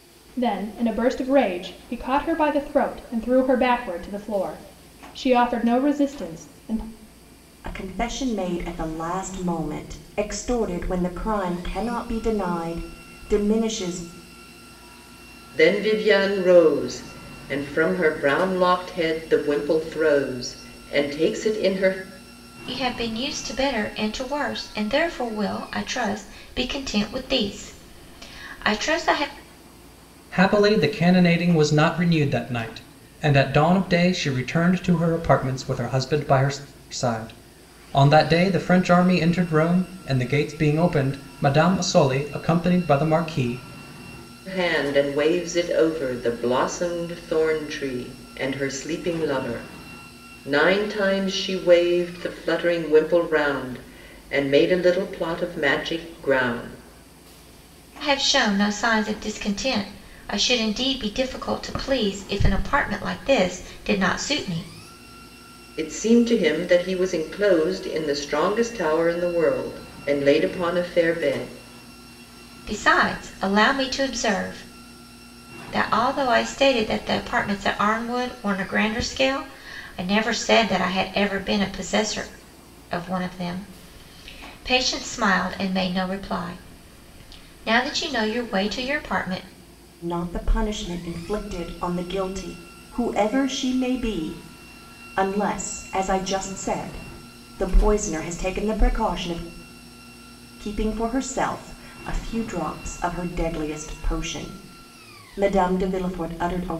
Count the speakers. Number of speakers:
5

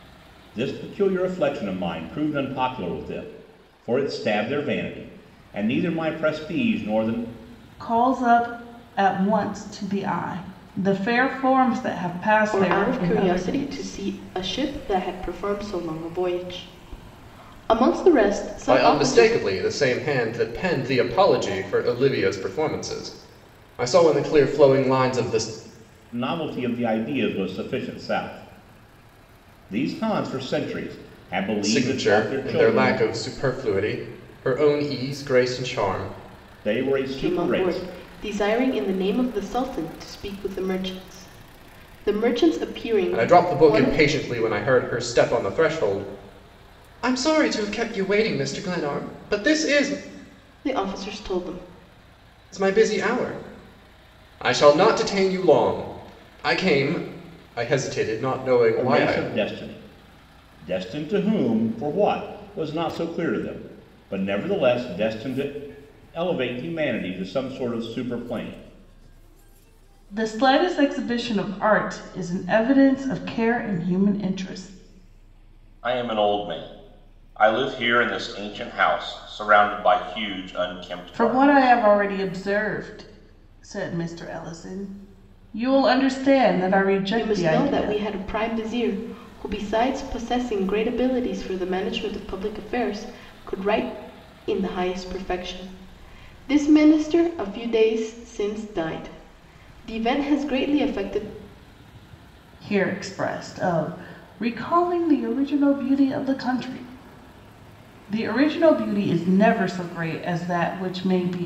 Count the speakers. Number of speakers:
4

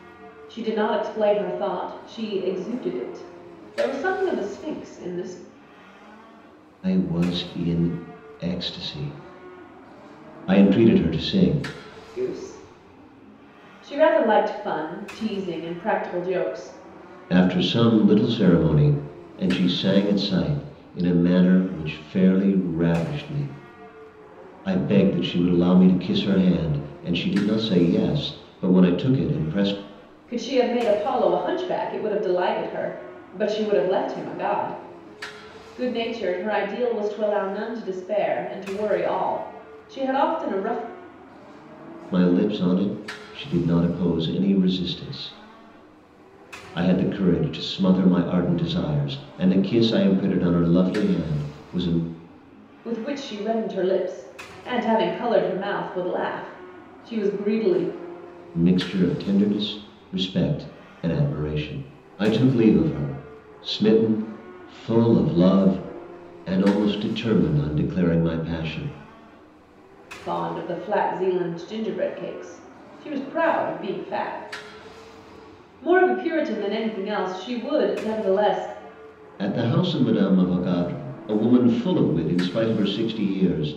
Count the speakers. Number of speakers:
2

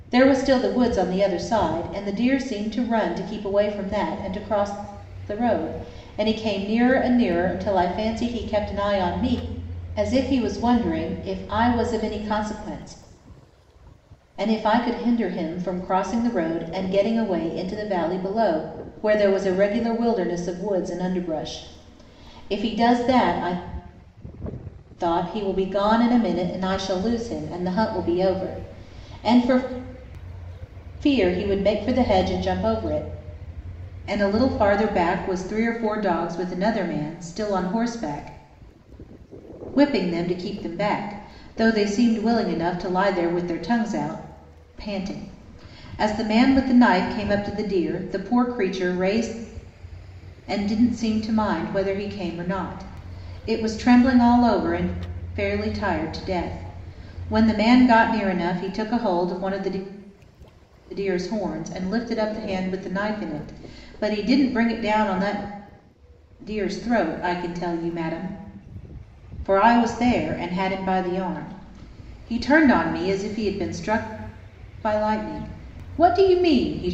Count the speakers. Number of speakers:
1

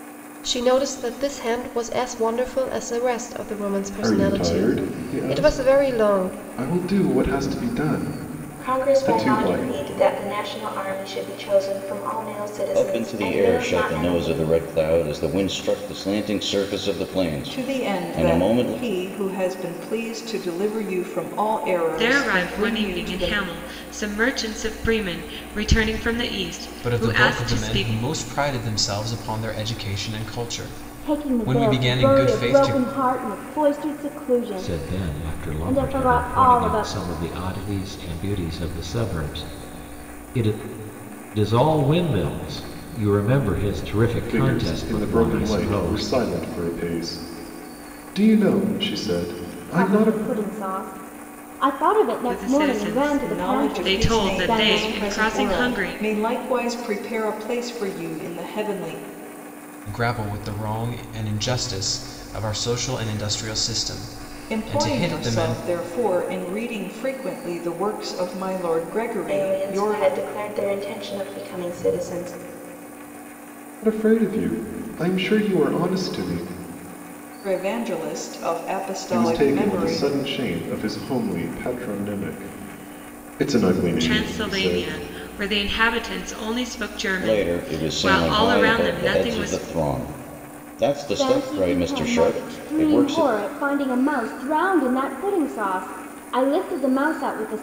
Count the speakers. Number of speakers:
9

